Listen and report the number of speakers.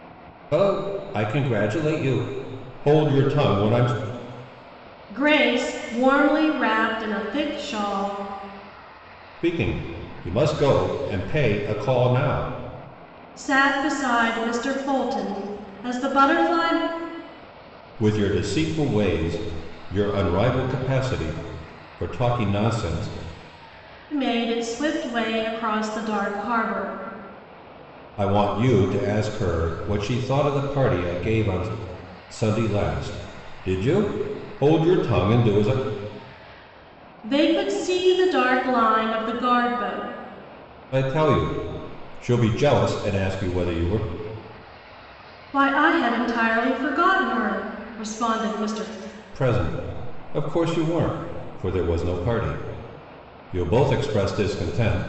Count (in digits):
2